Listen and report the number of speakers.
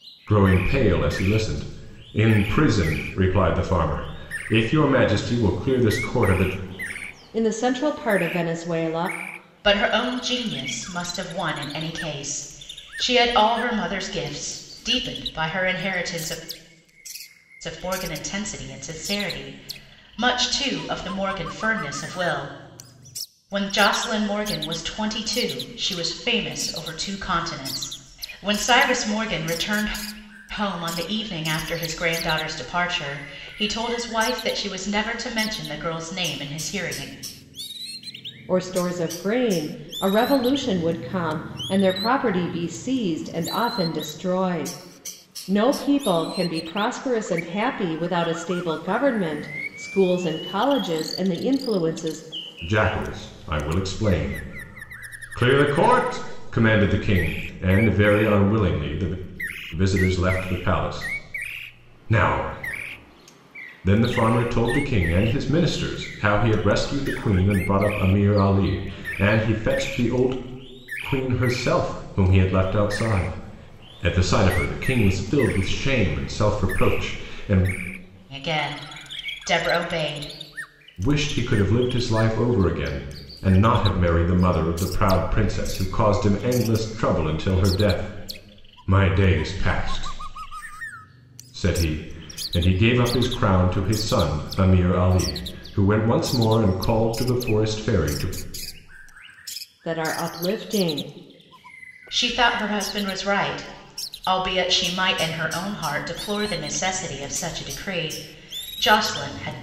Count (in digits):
3